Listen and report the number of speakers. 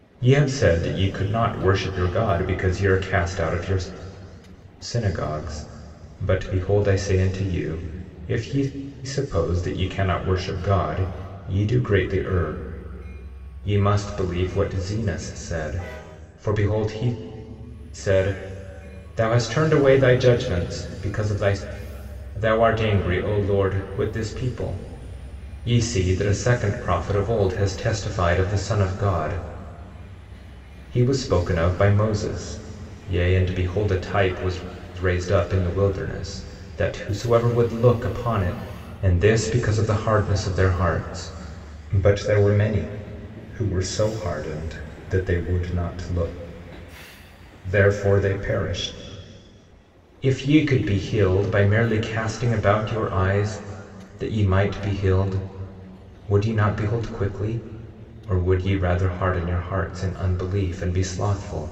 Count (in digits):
1